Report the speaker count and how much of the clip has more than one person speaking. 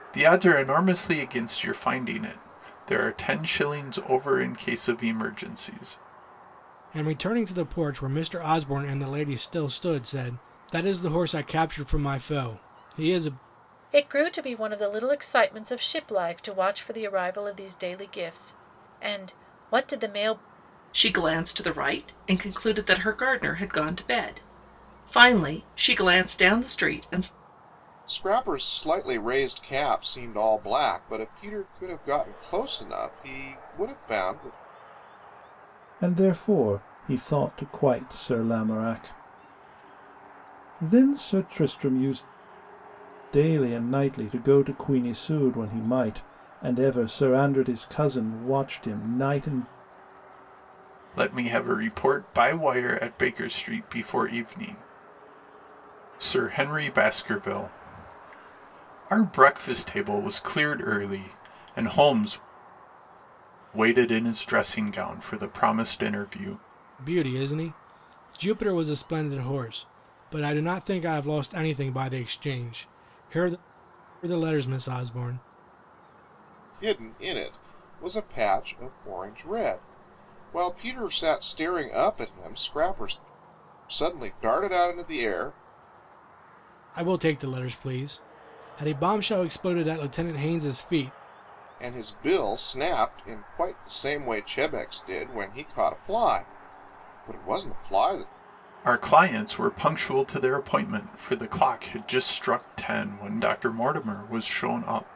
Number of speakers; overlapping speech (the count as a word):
six, no overlap